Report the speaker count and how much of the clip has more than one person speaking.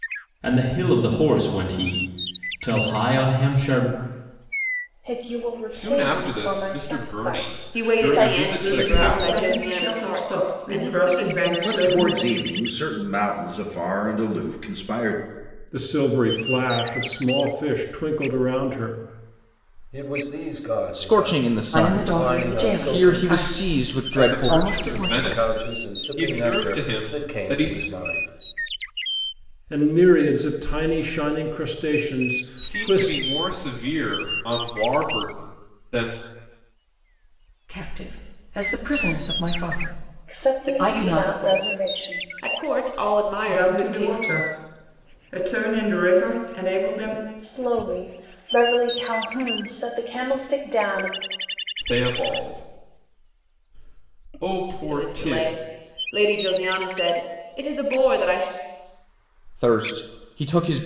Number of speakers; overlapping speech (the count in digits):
10, about 29%